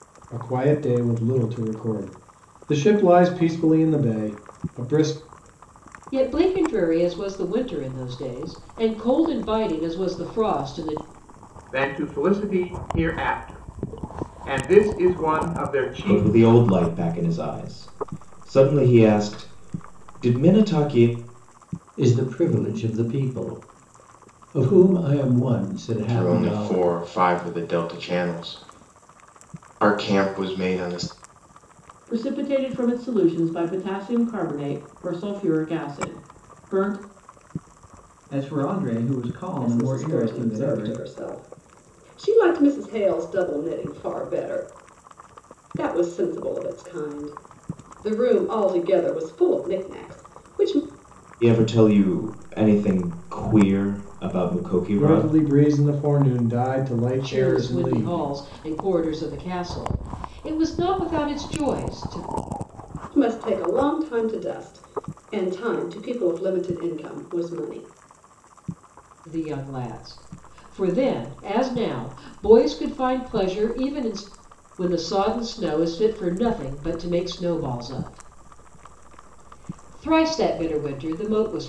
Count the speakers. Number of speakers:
9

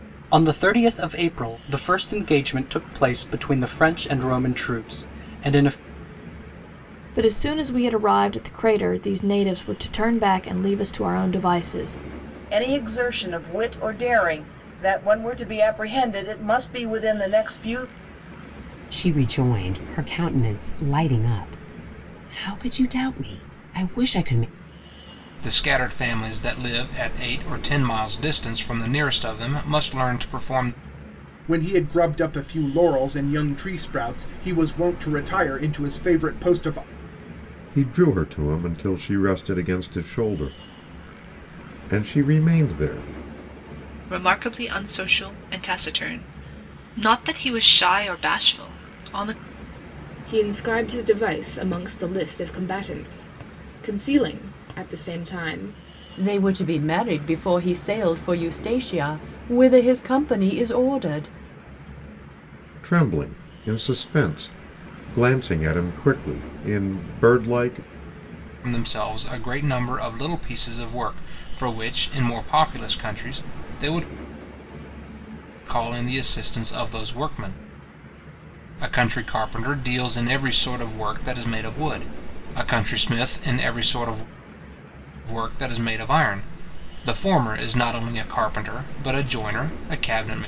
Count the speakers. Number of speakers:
10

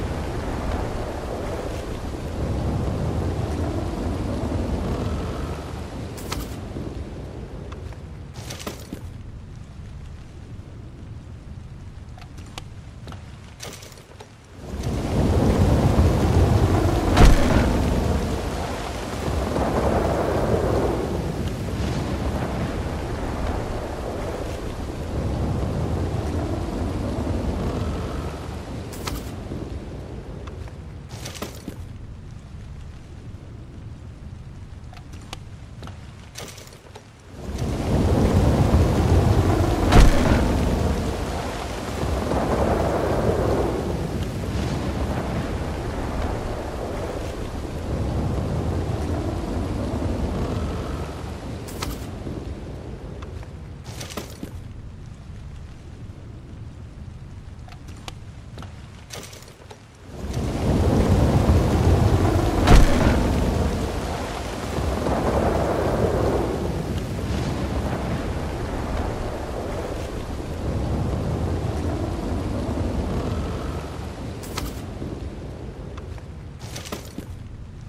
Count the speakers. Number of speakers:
0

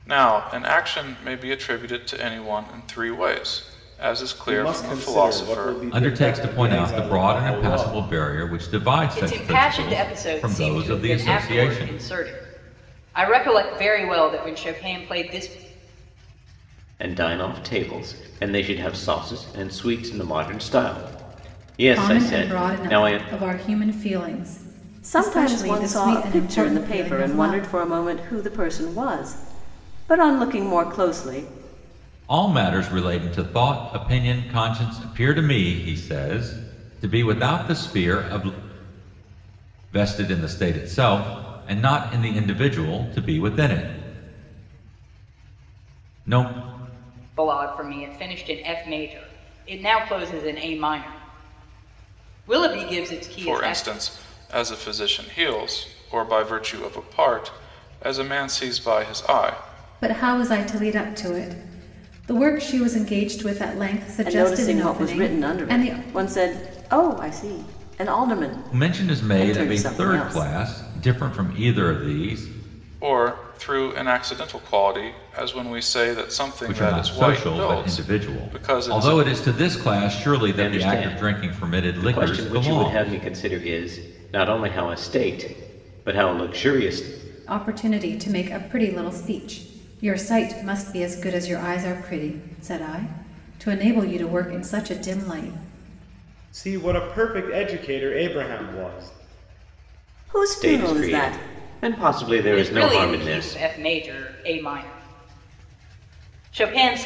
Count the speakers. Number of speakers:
7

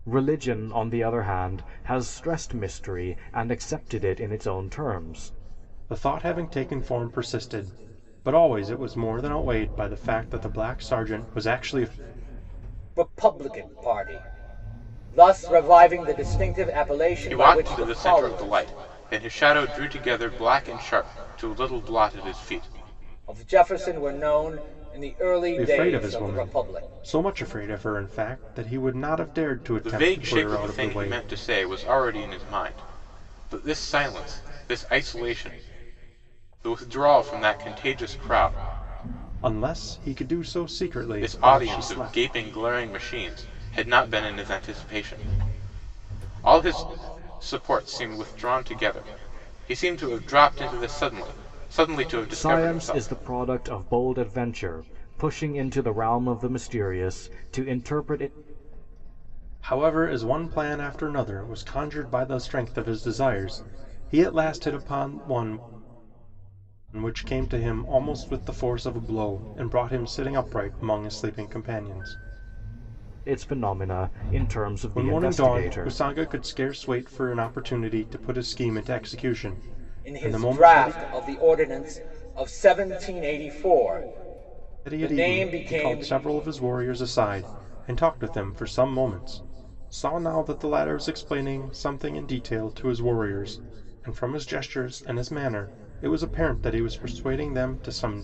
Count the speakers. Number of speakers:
4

